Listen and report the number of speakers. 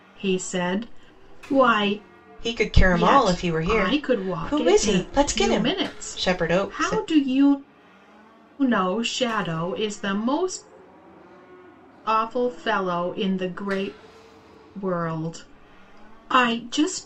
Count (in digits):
2